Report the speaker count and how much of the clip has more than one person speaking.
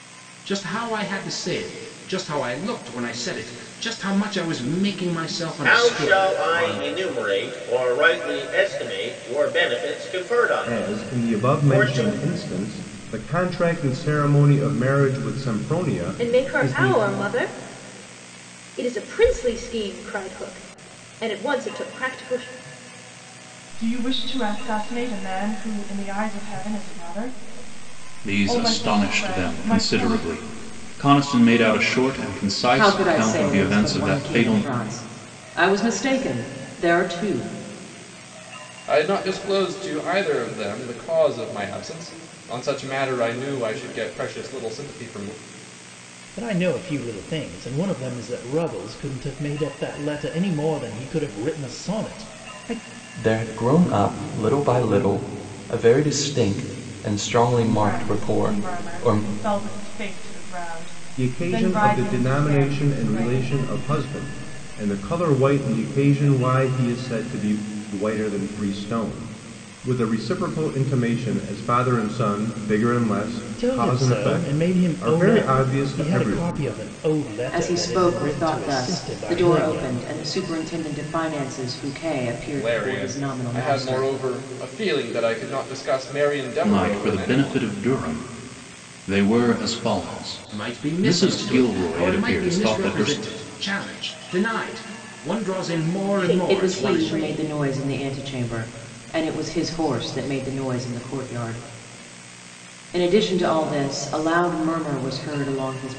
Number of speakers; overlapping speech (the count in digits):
10, about 23%